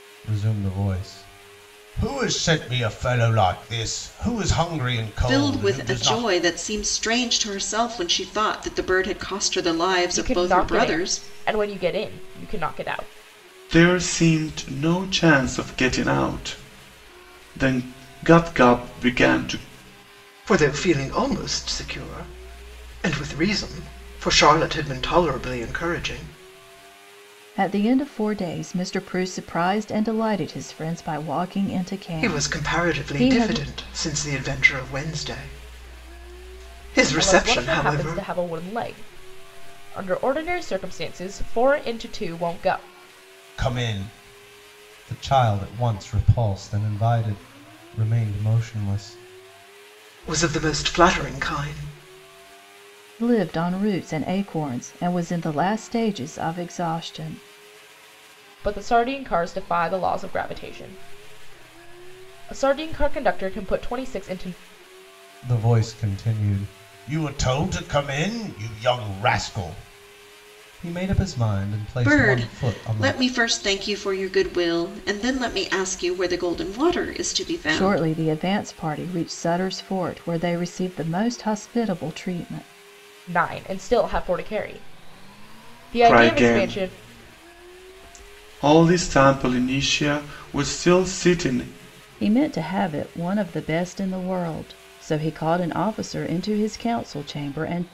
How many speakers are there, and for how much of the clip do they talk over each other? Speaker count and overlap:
six, about 8%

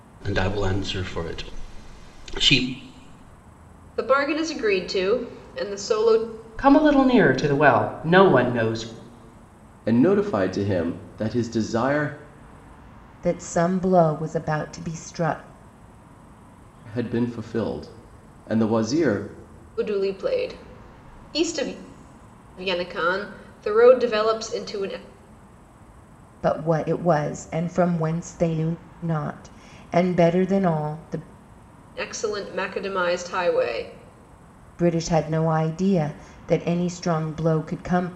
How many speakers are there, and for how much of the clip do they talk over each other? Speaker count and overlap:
five, no overlap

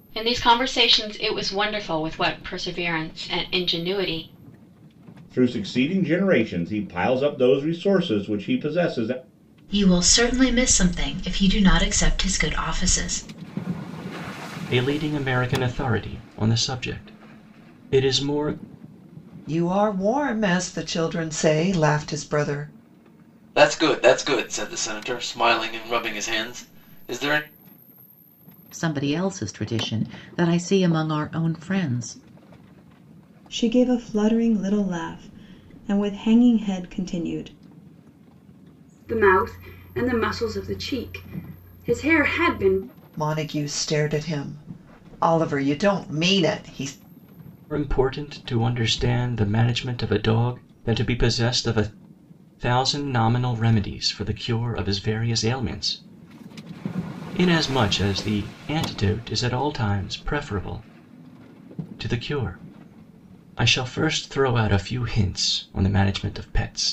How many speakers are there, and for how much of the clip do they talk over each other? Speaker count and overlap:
nine, no overlap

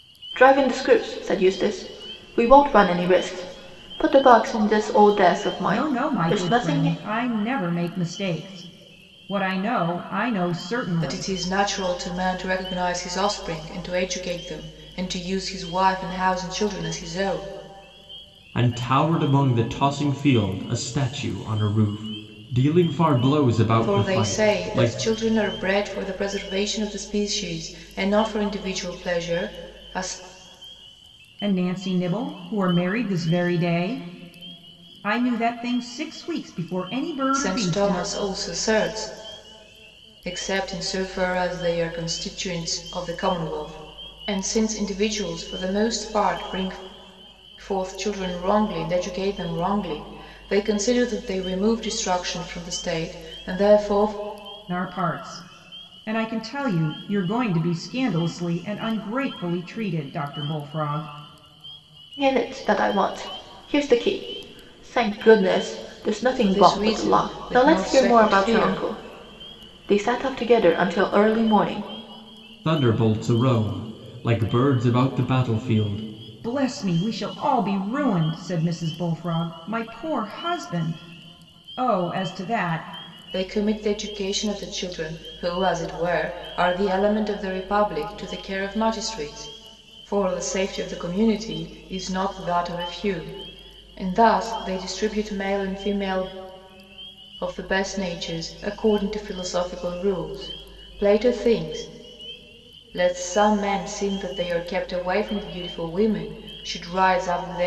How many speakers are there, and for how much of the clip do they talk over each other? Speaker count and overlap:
four, about 6%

